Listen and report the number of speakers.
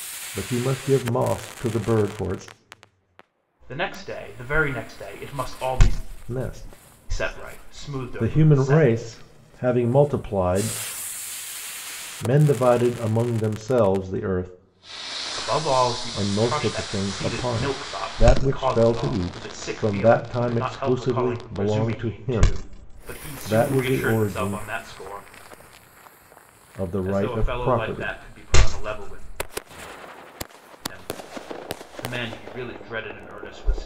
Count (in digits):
2